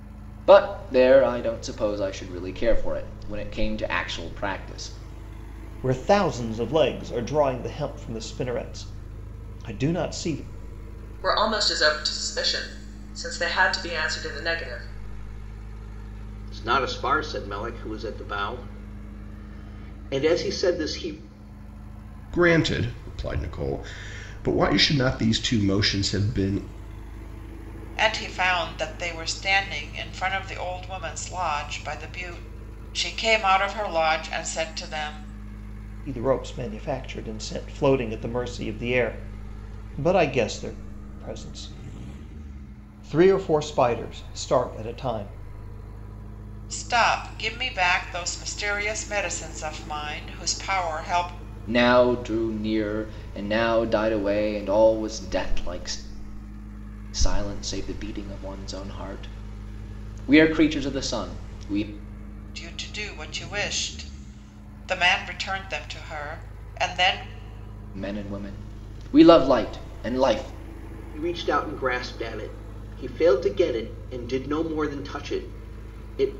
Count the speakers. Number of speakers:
six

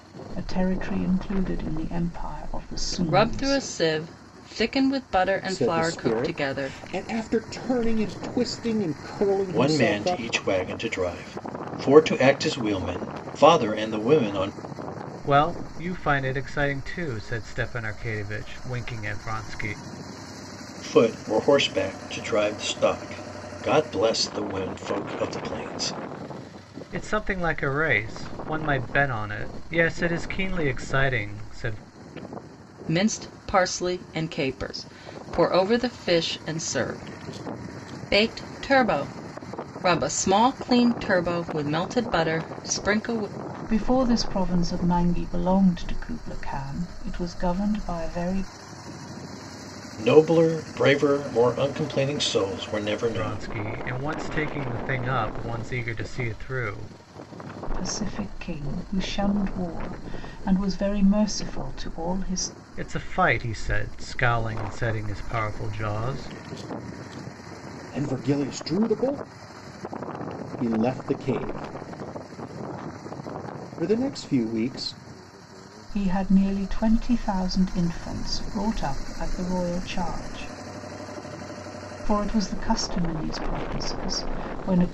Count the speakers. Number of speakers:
five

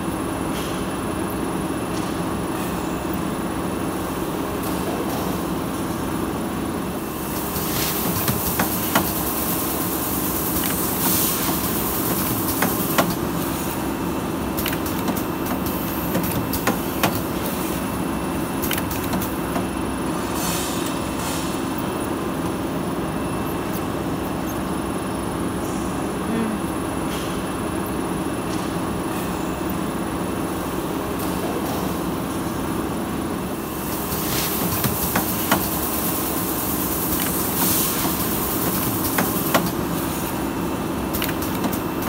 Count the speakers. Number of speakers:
zero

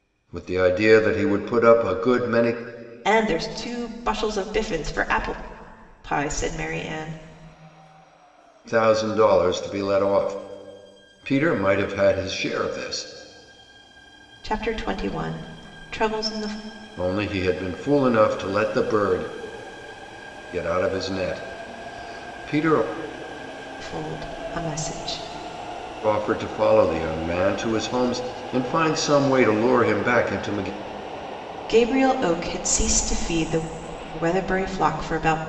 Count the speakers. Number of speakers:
two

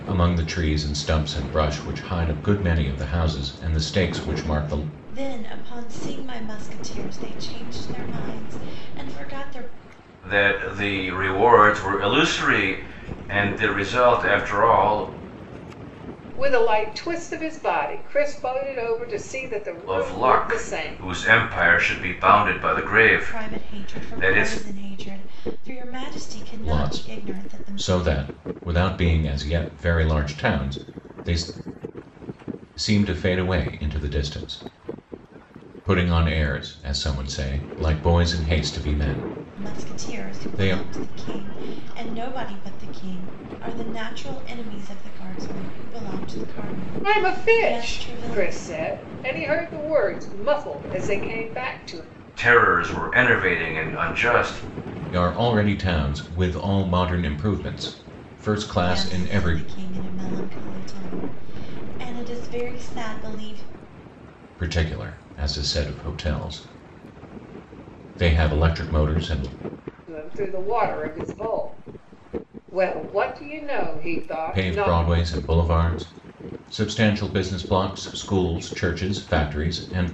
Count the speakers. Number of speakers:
four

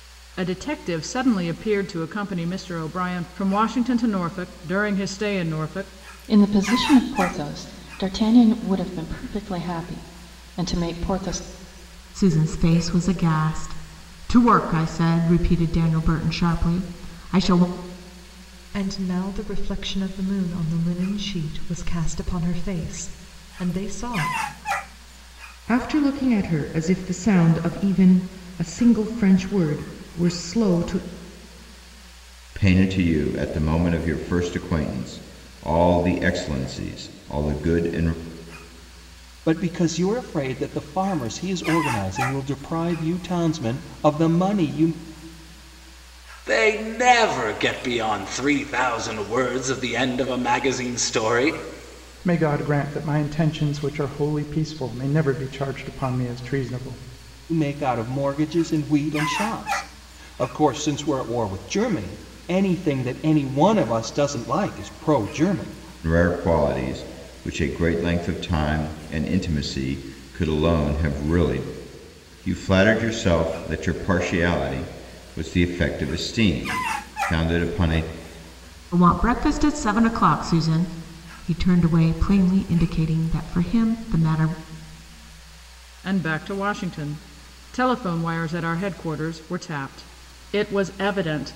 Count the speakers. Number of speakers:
nine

